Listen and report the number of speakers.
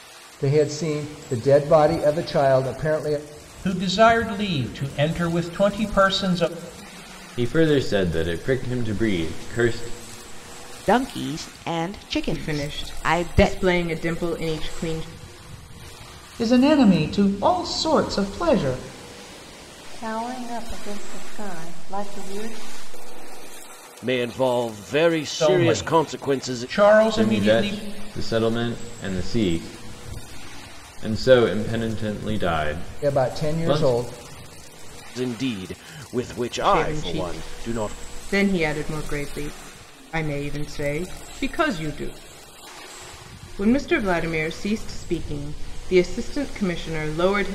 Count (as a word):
eight